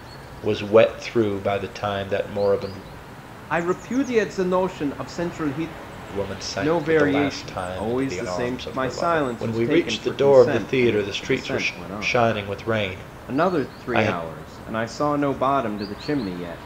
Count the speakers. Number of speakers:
2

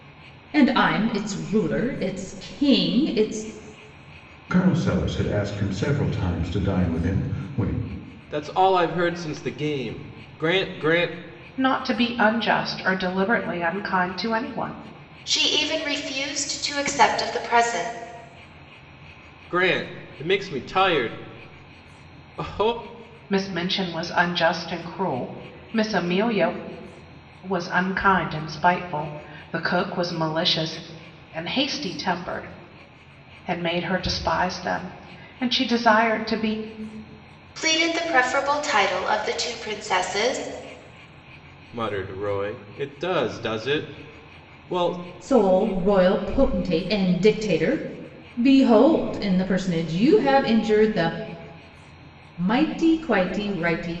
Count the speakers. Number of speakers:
5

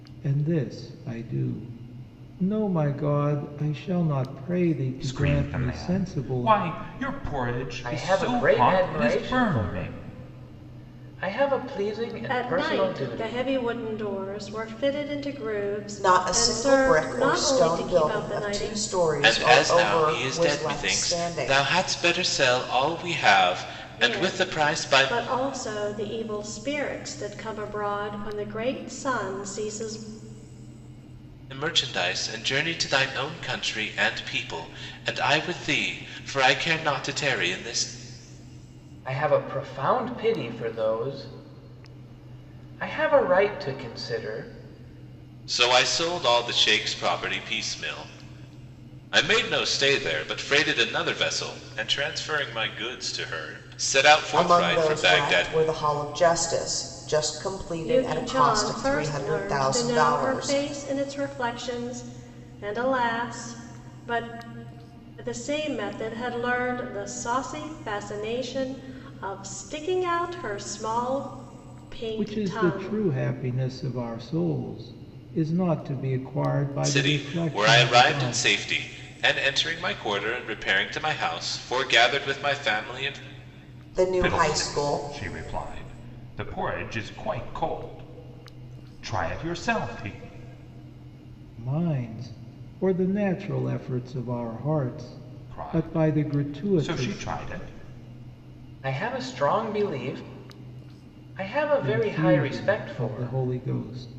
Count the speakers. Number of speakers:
6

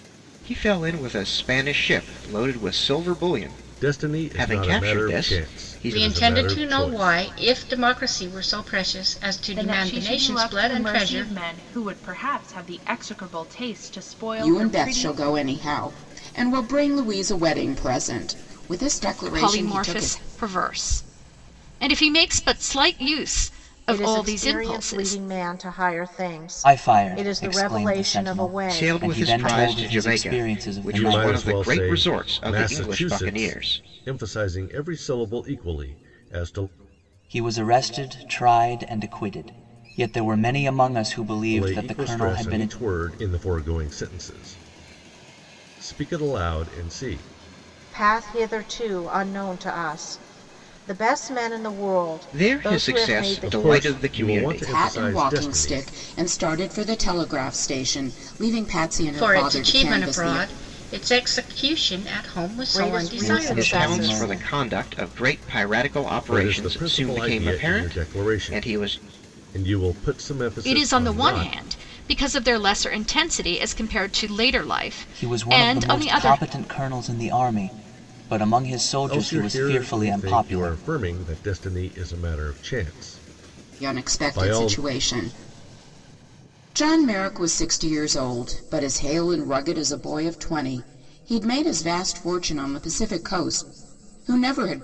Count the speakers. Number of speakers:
8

